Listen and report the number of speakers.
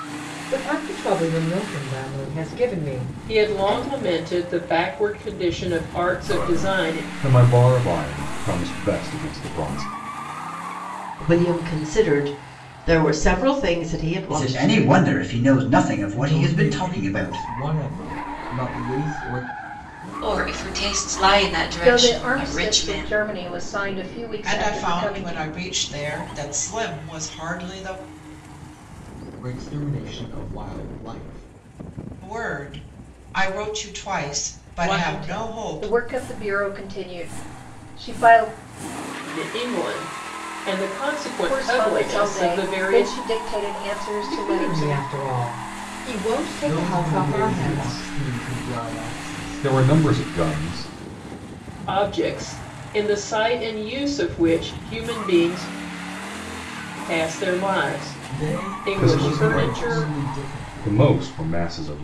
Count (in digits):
9